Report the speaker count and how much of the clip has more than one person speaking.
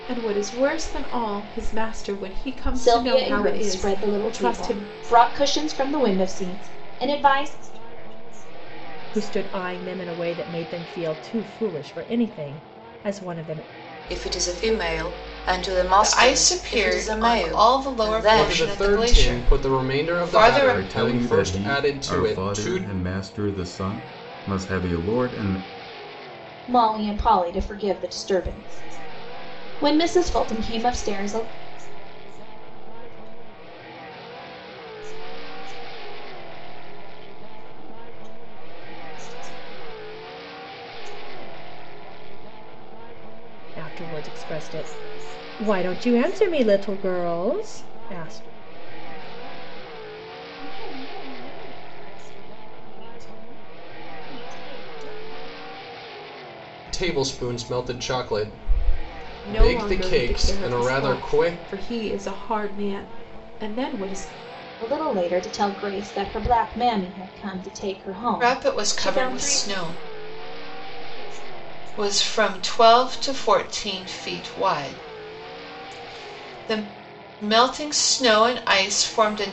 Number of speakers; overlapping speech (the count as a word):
eight, about 32%